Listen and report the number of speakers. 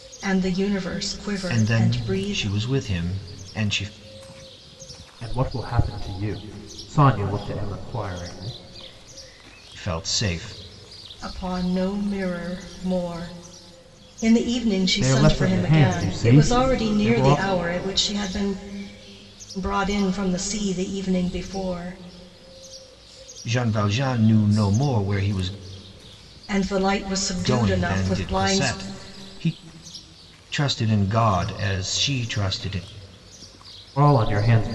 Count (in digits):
3